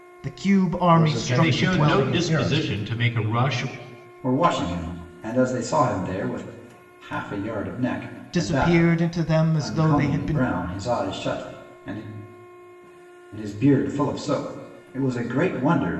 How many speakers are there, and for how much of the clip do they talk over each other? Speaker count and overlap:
4, about 21%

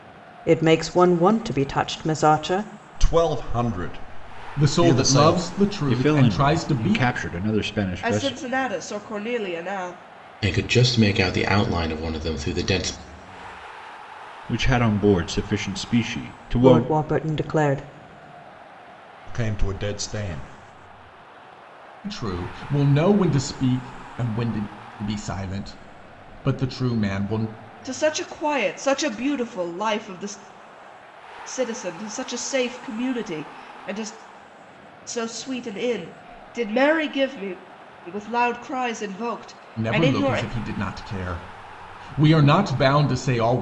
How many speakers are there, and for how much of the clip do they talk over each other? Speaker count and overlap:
6, about 8%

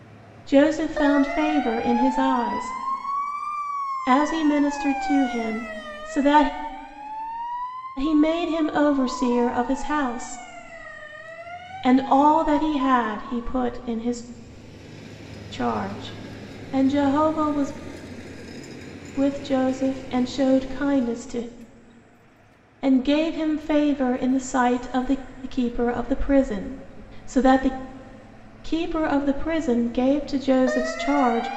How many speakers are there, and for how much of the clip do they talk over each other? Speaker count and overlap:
1, no overlap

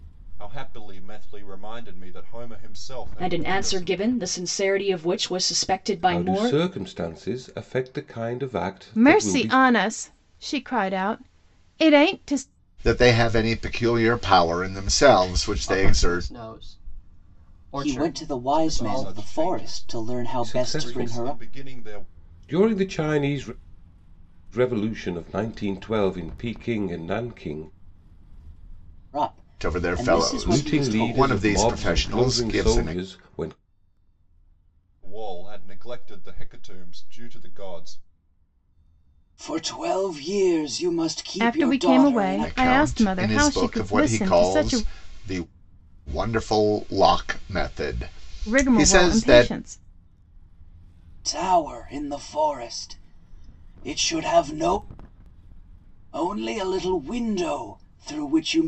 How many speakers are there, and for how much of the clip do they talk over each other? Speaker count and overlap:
7, about 26%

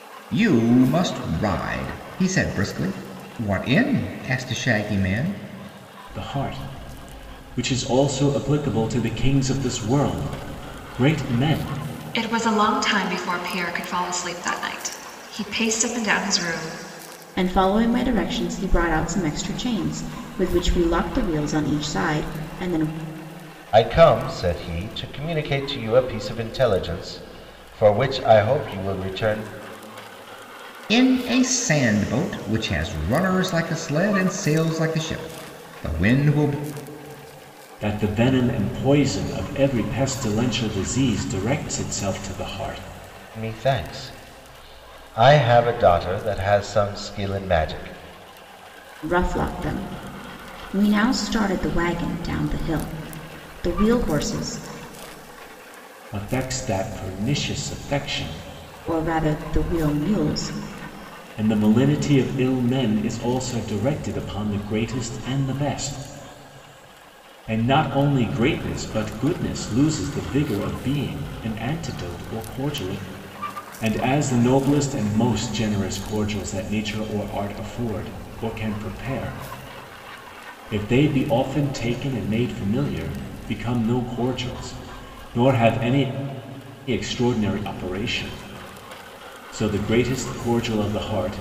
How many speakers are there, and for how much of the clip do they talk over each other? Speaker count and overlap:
5, no overlap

